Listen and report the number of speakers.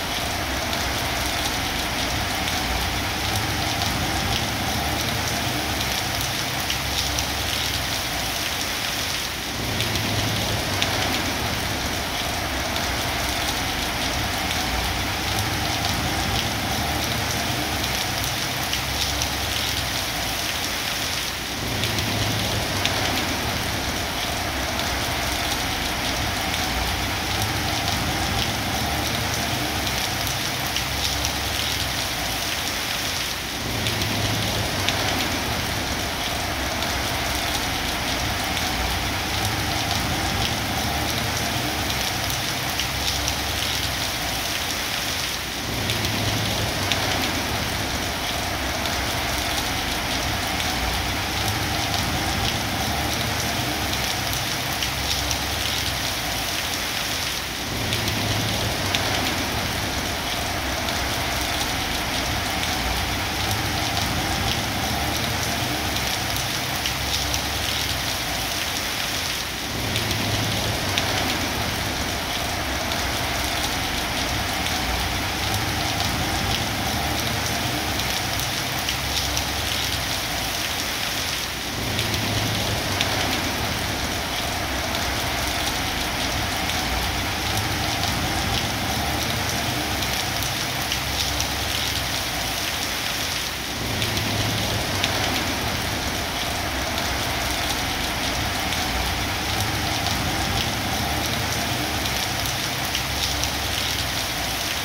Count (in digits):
0